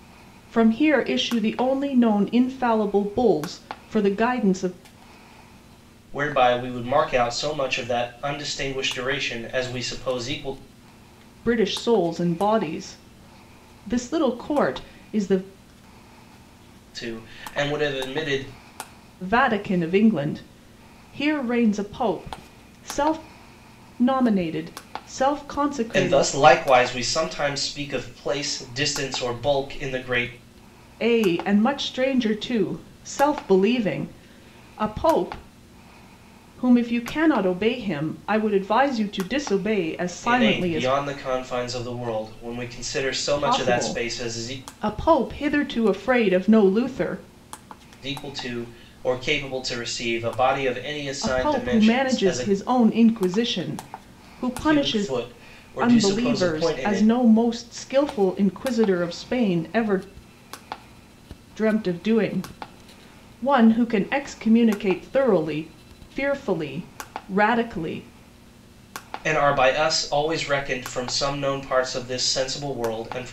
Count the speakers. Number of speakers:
2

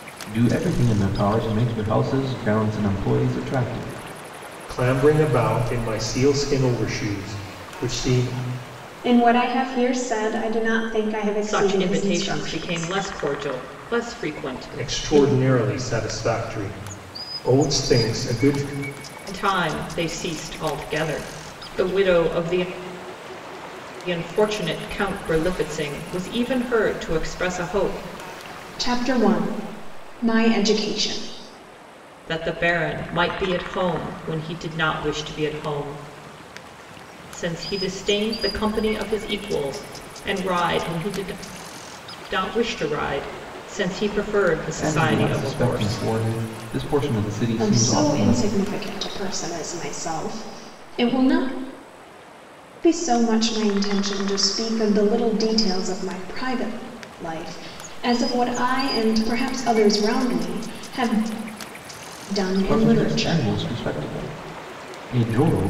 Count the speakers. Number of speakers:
4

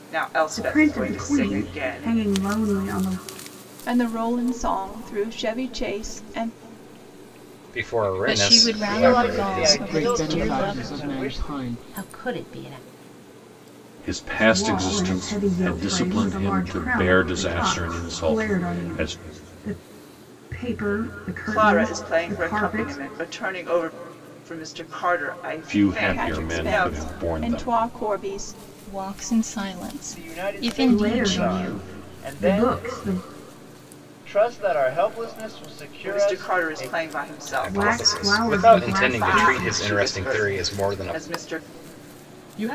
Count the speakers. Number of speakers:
9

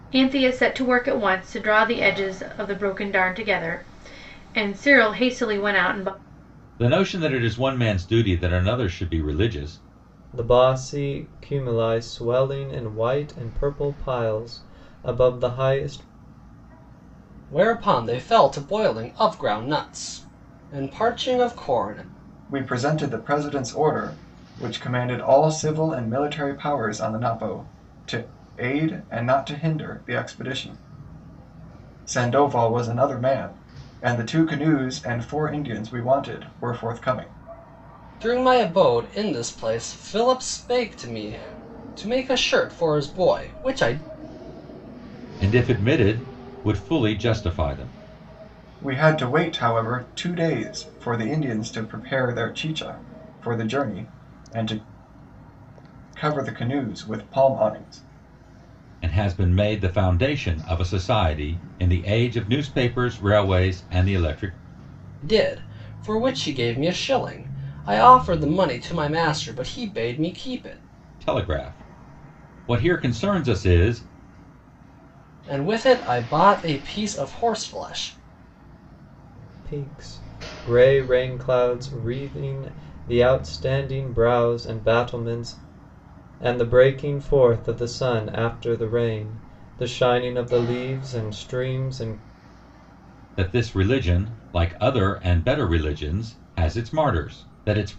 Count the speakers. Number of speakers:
5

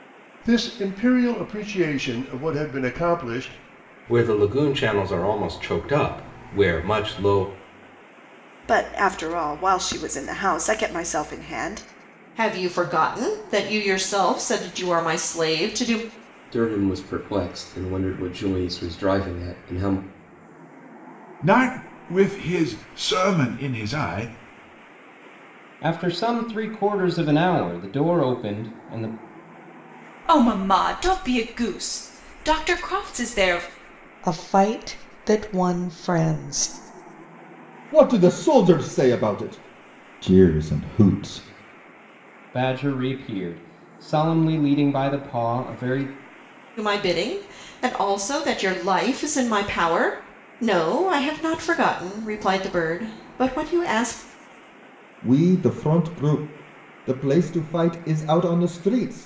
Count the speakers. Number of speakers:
10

